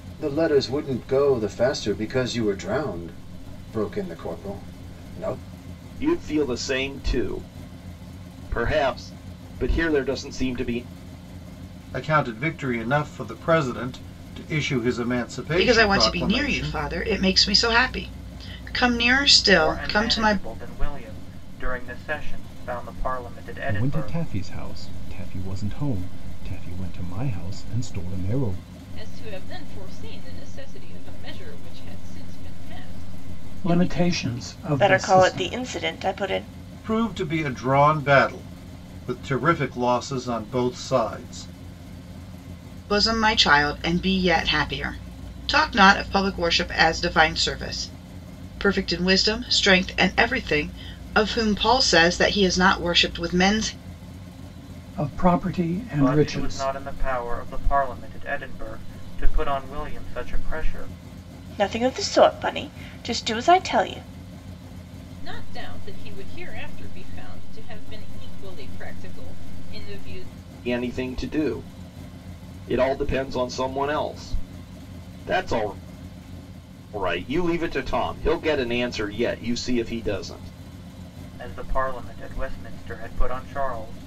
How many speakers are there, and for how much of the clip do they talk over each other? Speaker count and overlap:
9, about 6%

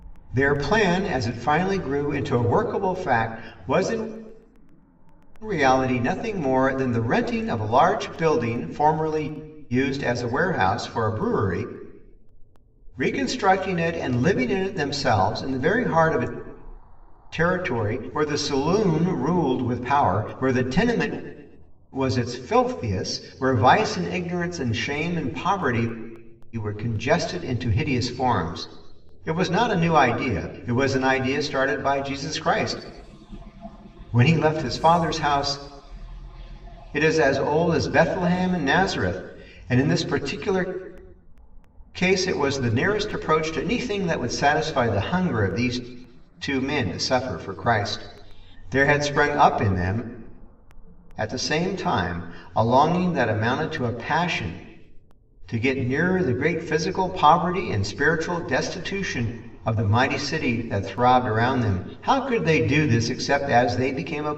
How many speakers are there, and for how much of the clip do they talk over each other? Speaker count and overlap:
1, no overlap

